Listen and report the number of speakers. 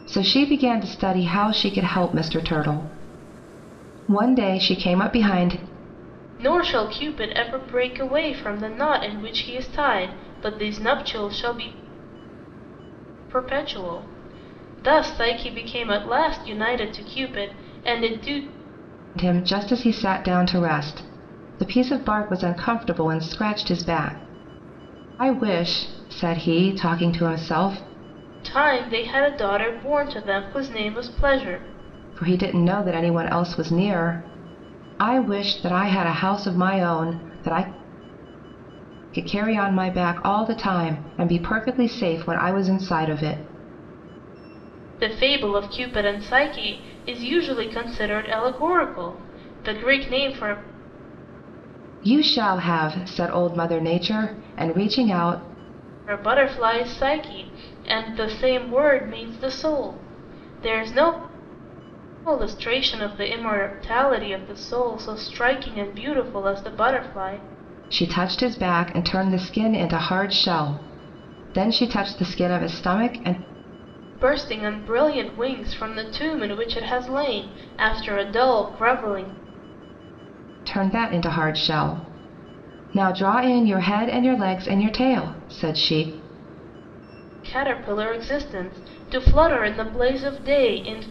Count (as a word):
two